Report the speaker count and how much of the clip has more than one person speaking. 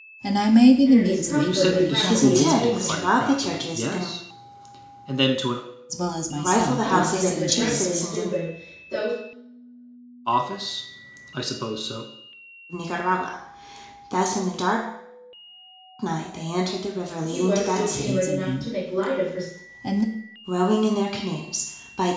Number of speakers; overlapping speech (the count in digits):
4, about 34%